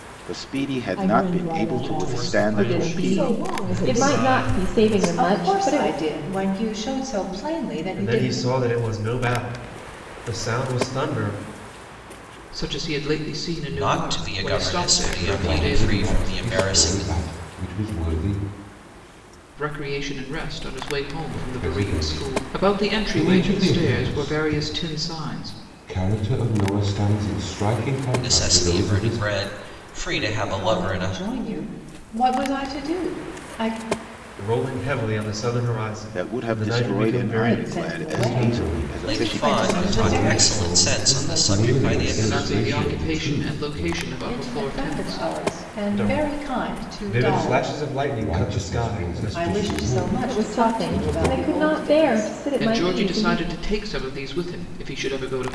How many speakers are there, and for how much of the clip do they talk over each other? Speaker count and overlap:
9, about 53%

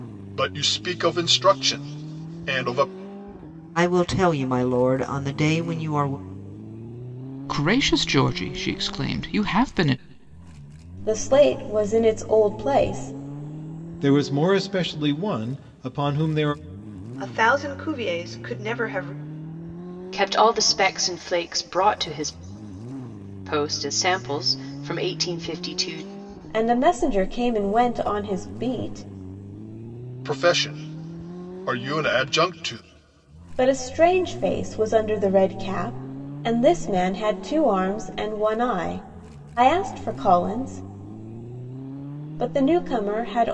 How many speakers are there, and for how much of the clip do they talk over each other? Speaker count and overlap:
7, no overlap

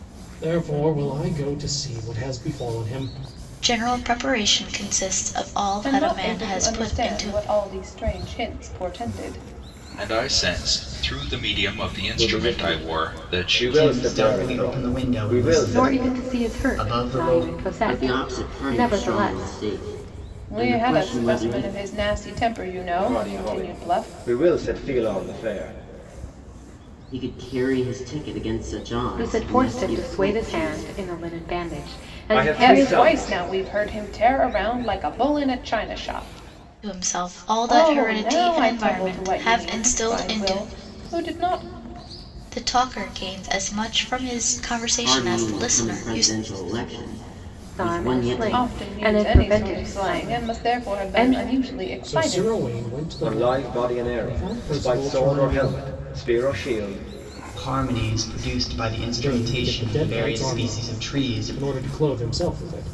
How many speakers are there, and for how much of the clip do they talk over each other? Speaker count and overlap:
8, about 44%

